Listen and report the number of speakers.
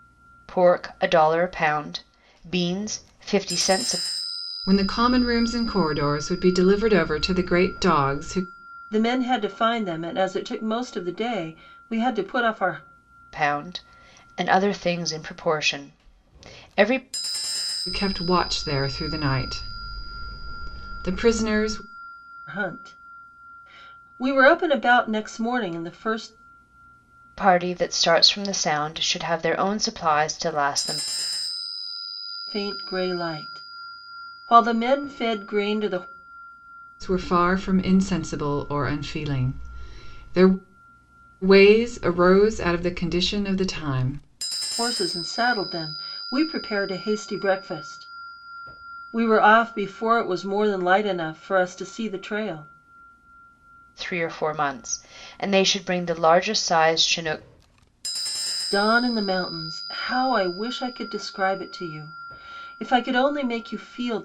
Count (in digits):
3